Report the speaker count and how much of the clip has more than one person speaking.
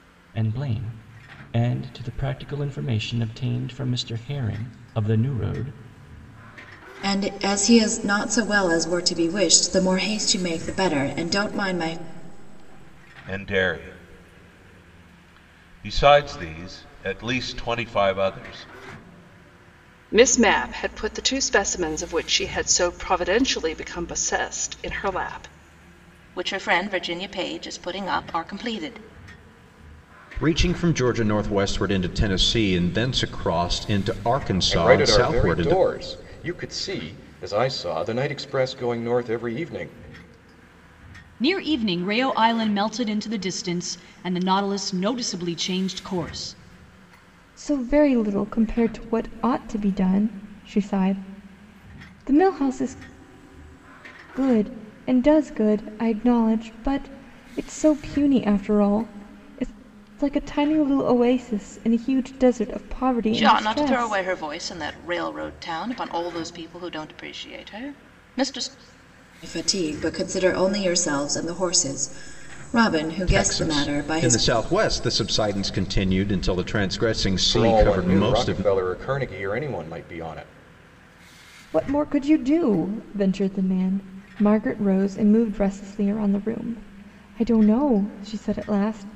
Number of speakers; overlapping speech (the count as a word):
nine, about 5%